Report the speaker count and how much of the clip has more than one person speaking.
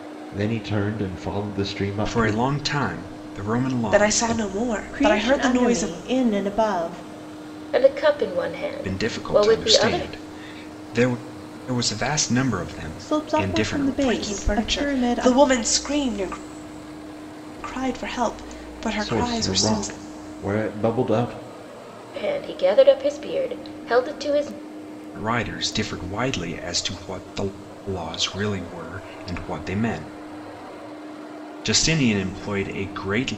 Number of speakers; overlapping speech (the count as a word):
five, about 21%